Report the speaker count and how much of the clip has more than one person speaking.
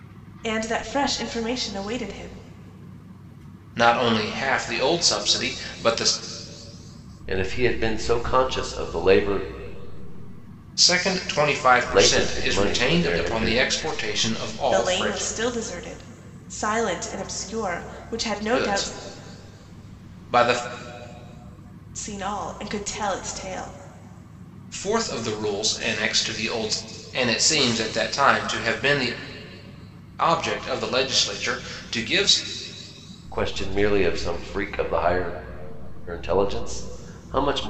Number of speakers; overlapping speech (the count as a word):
three, about 8%